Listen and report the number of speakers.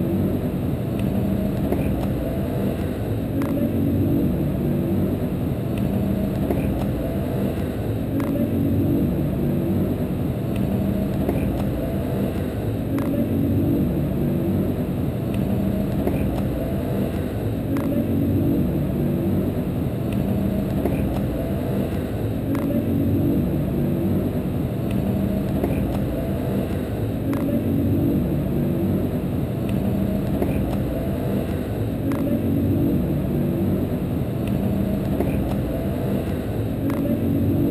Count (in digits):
0